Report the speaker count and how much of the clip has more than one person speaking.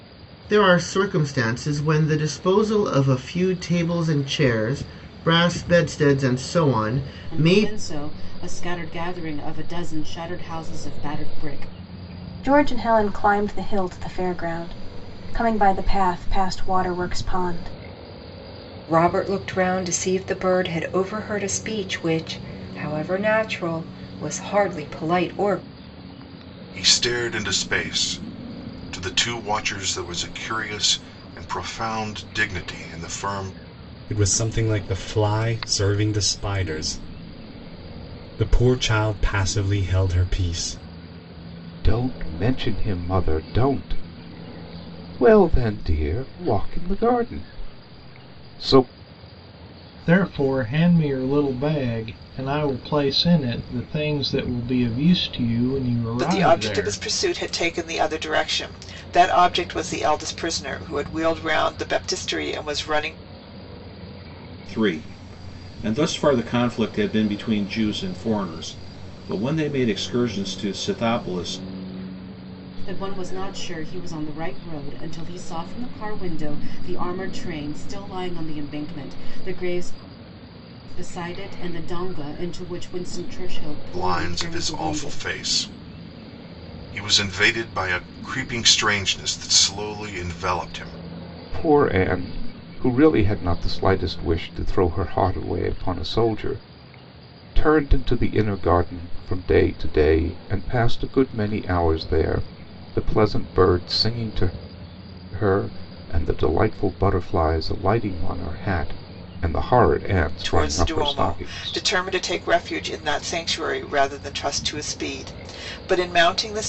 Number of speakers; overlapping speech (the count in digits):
10, about 3%